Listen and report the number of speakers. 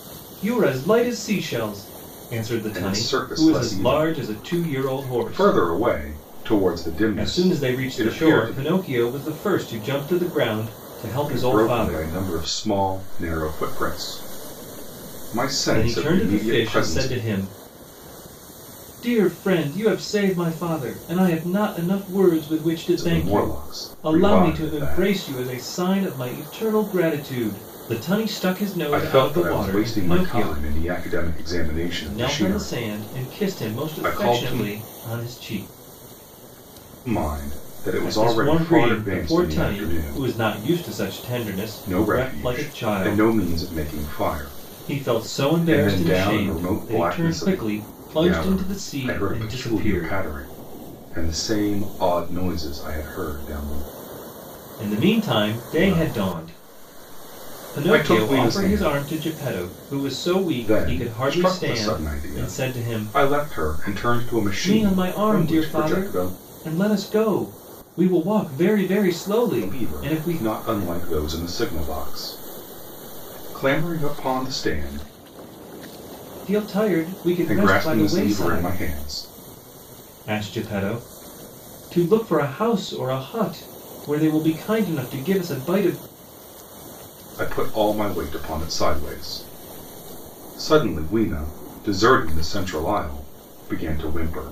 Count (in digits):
2